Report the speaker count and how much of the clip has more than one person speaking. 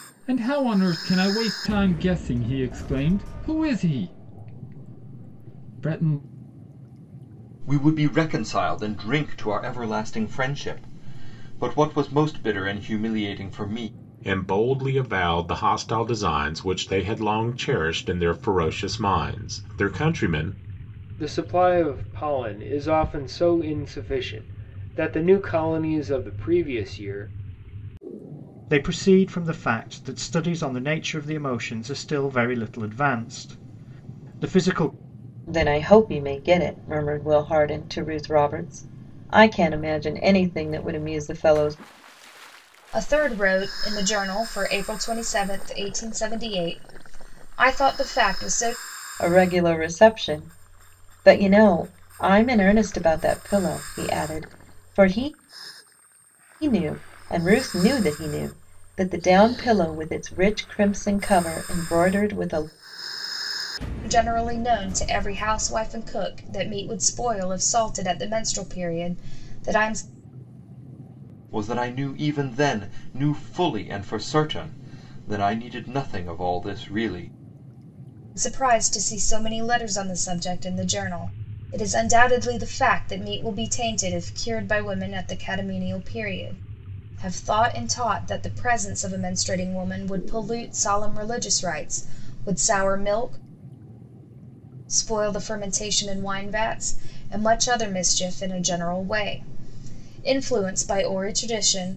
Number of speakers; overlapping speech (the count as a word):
seven, no overlap